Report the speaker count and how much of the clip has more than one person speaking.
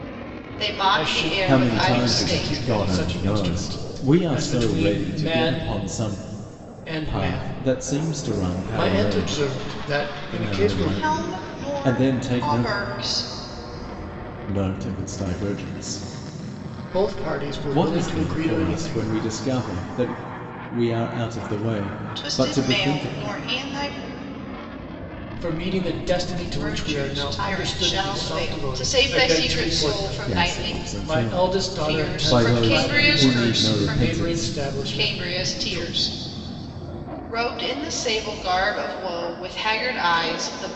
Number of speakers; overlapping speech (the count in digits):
3, about 48%